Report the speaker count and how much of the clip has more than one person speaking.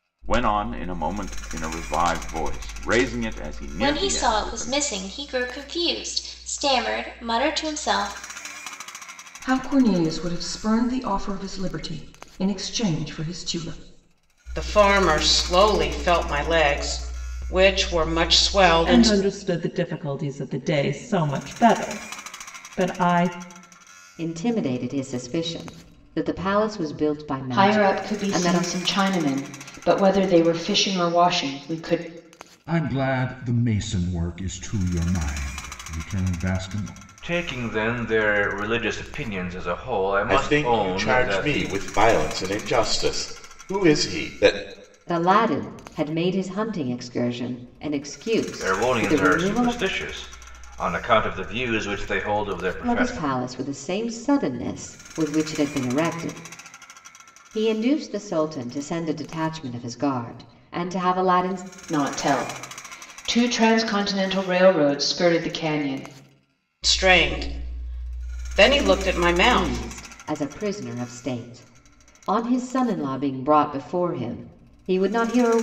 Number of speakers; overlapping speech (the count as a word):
ten, about 8%